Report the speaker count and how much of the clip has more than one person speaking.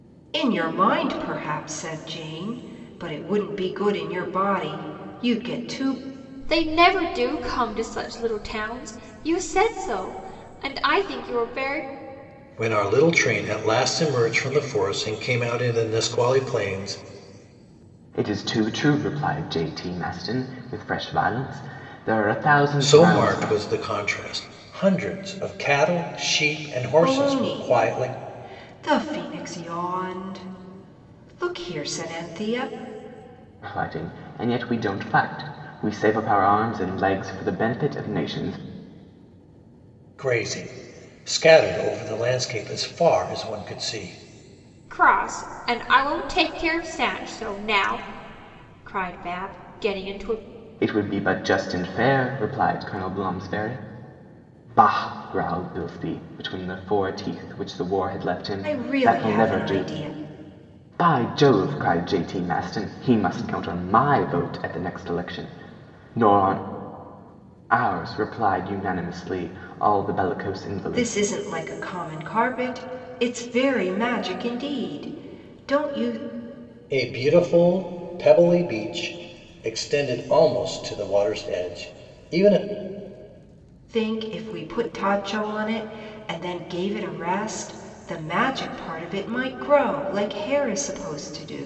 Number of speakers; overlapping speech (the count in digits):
4, about 4%